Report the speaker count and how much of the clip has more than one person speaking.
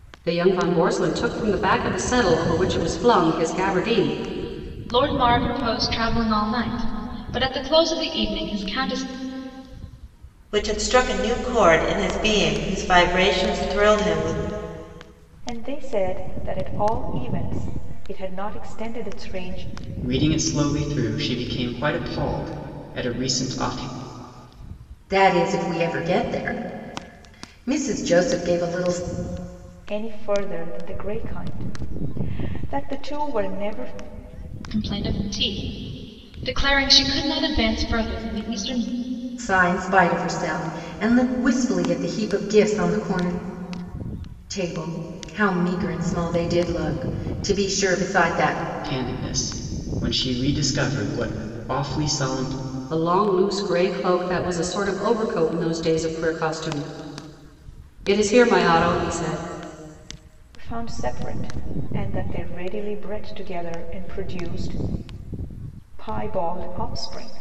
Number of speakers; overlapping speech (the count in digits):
6, no overlap